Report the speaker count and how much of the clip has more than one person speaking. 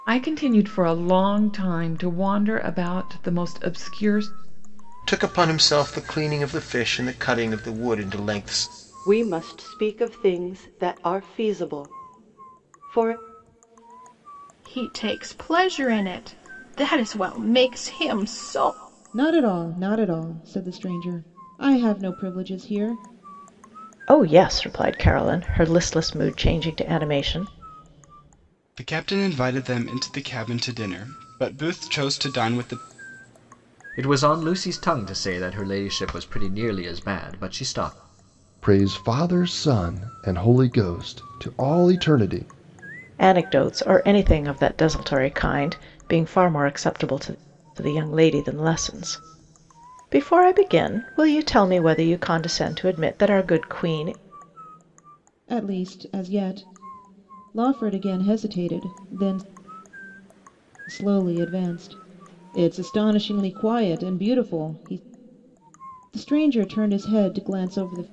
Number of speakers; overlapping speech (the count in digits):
9, no overlap